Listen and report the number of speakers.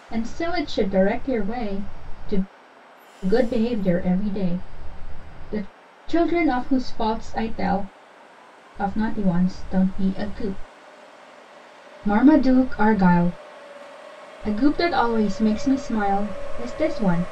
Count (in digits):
1